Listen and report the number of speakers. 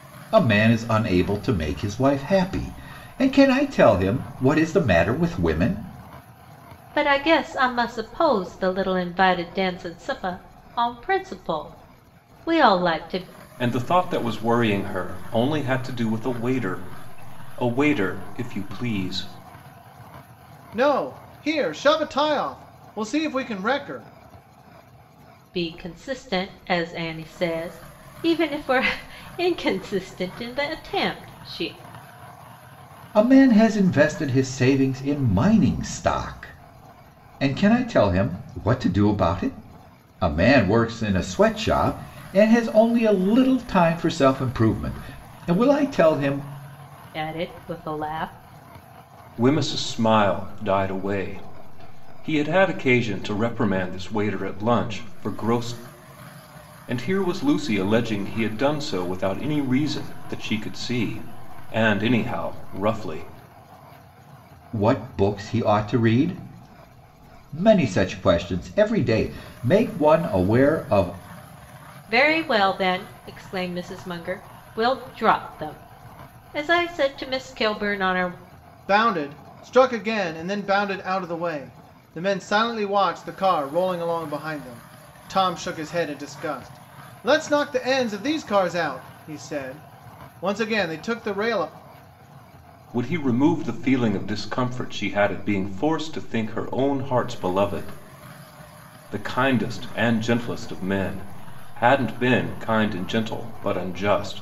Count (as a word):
four